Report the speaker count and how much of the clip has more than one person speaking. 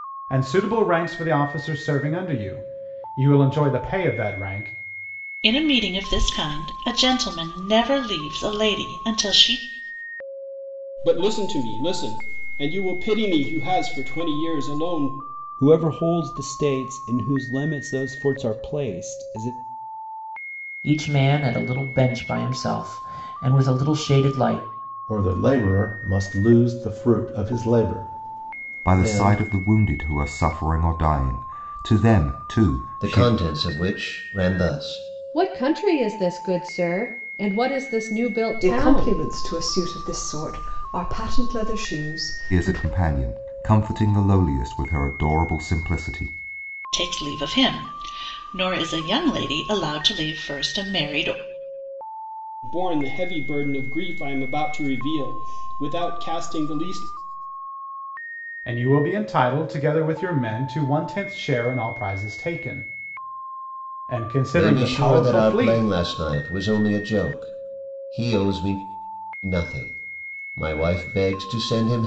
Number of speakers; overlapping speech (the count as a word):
ten, about 5%